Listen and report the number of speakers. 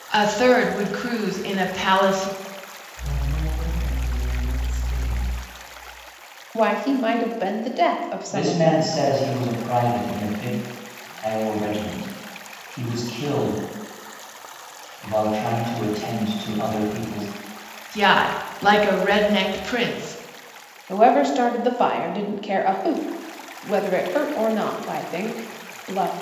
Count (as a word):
four